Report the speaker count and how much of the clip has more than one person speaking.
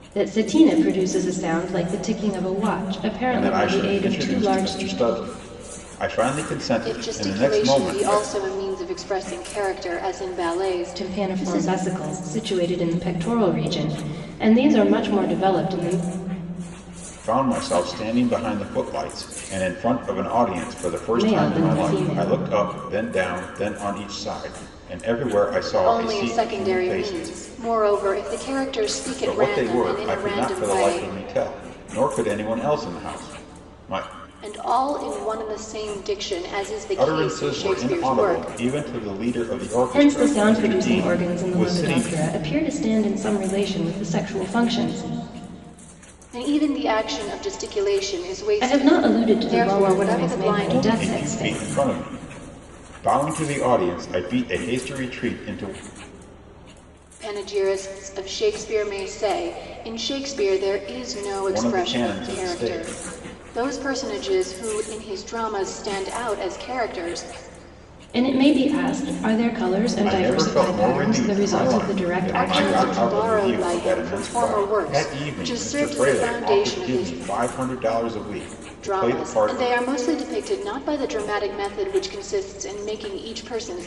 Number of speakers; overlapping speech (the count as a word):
three, about 30%